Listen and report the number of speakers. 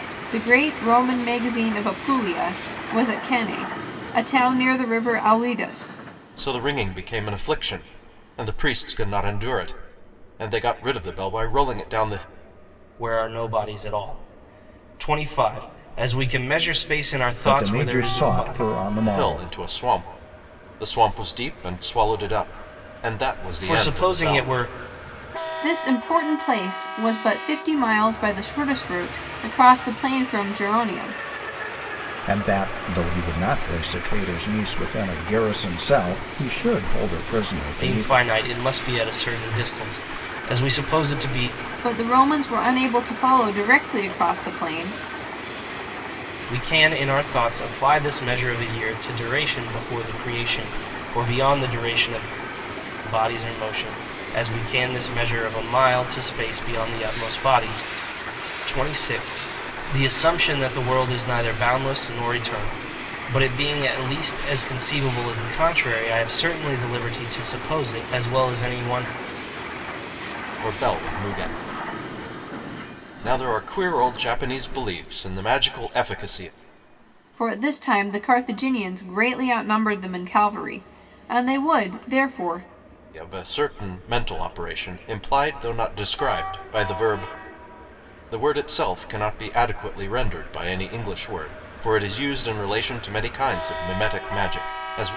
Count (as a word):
four